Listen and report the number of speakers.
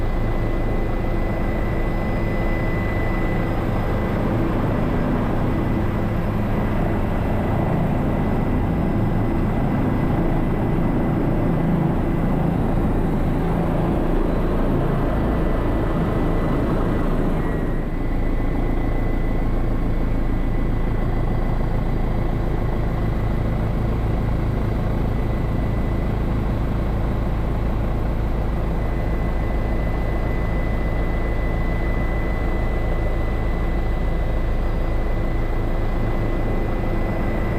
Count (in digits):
0